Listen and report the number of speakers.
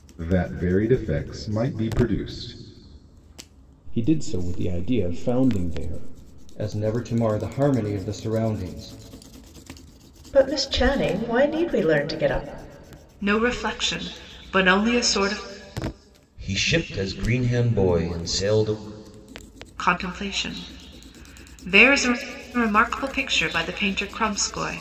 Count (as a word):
six